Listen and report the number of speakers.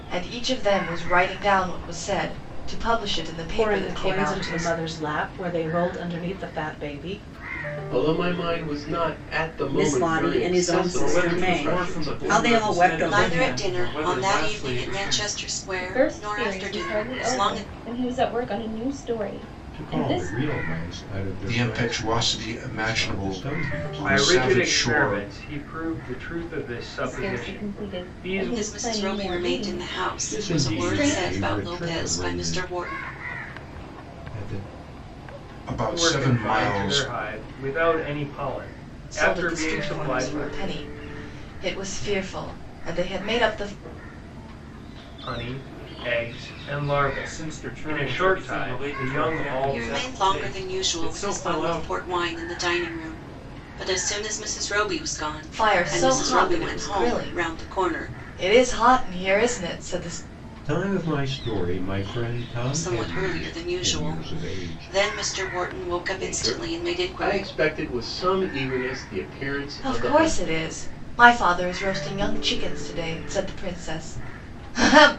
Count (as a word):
ten